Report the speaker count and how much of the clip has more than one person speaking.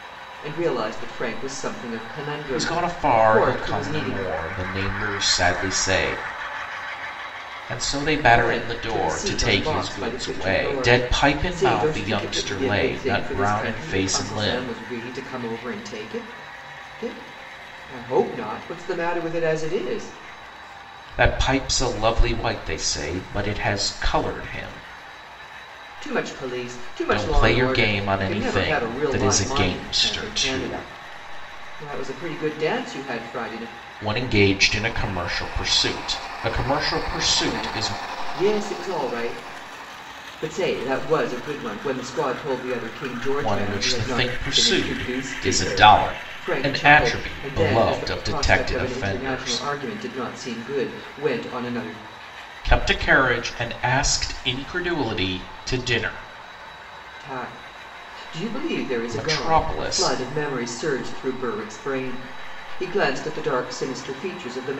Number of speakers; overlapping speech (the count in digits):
2, about 30%